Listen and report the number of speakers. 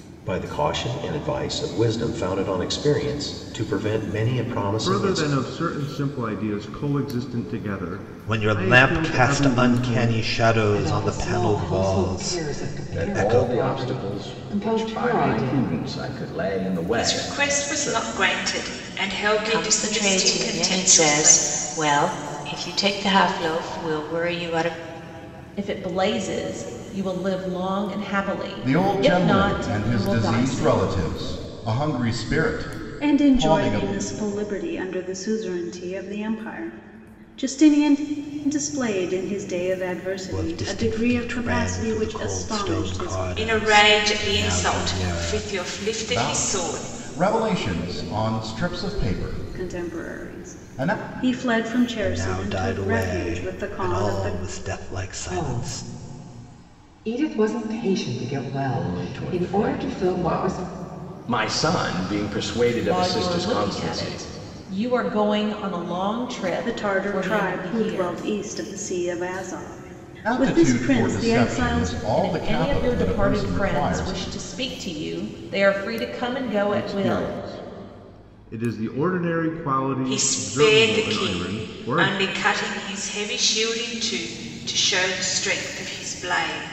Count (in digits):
10